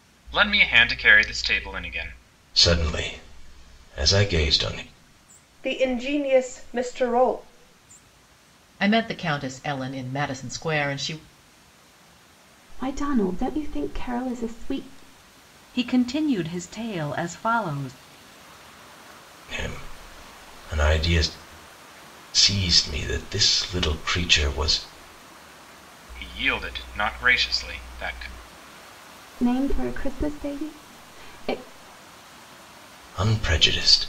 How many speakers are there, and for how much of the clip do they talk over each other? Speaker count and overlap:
six, no overlap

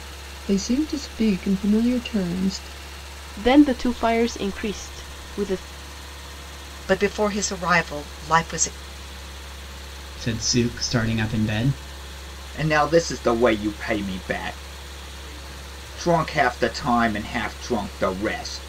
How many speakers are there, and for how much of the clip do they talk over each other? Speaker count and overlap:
five, no overlap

